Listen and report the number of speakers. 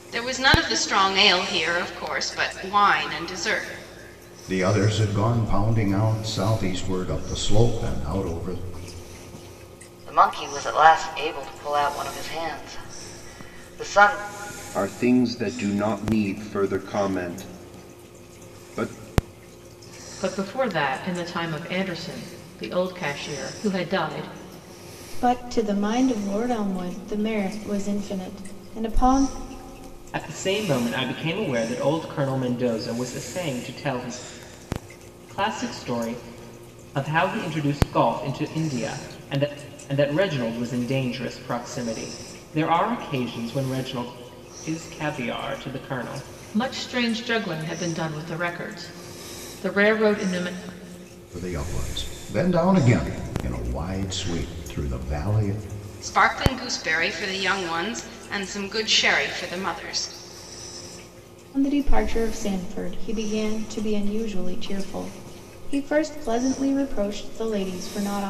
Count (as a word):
seven